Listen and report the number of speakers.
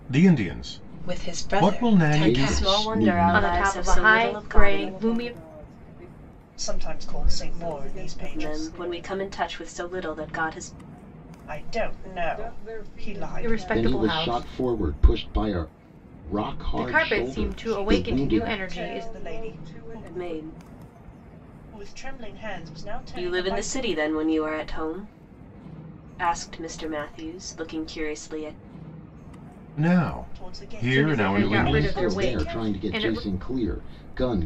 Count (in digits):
7